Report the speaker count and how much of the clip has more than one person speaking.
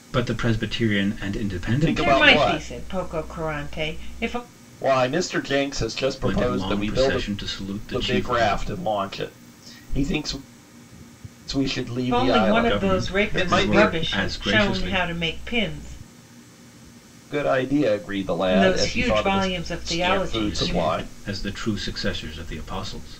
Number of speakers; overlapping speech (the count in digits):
3, about 34%